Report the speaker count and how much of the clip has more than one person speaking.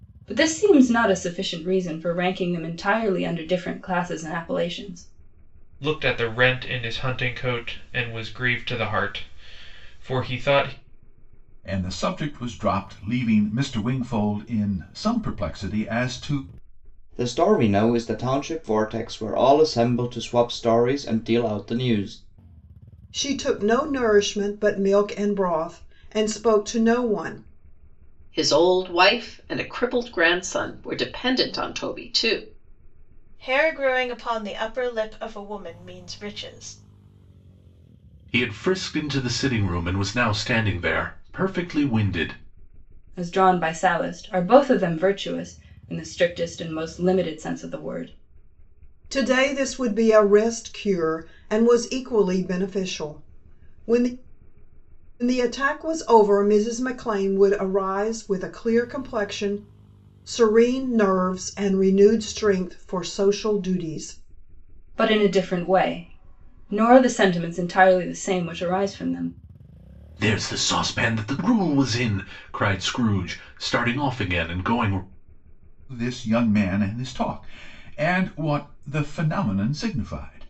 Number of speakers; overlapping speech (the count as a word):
eight, no overlap